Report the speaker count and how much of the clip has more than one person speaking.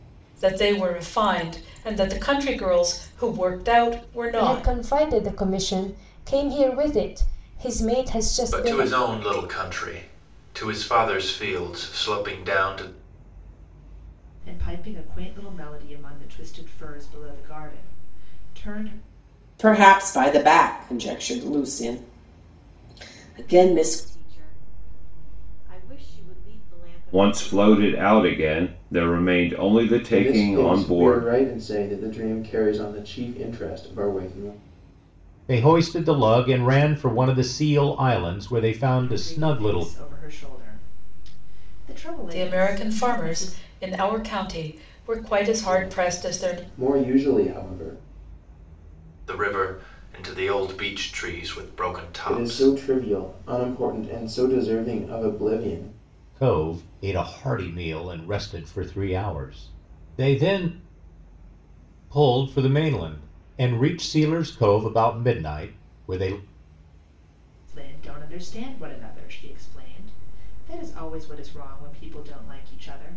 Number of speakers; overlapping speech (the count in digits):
9, about 10%